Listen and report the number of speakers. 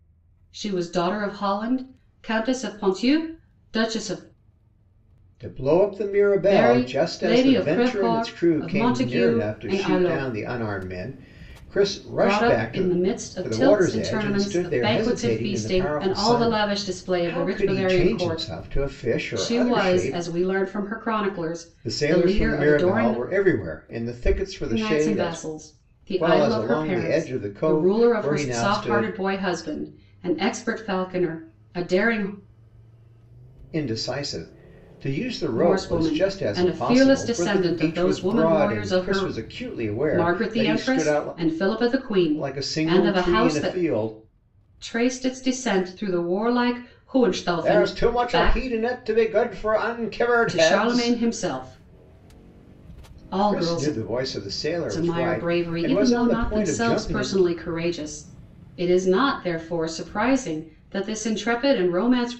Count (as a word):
two